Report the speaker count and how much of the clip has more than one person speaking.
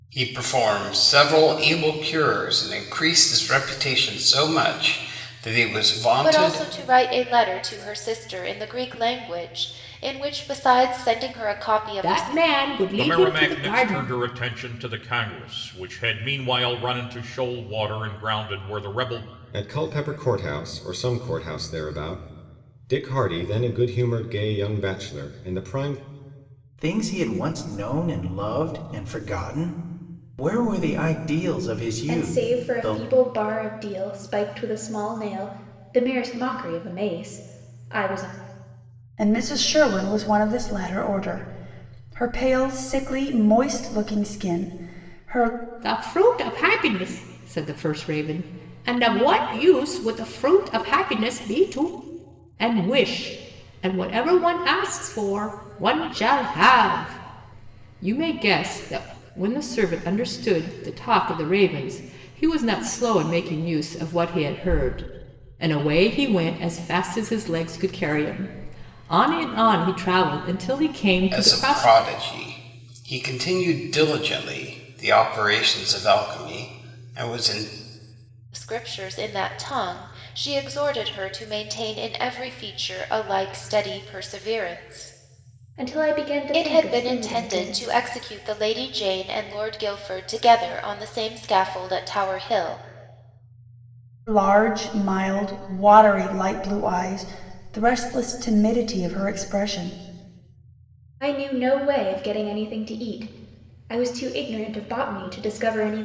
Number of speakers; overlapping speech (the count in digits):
8, about 5%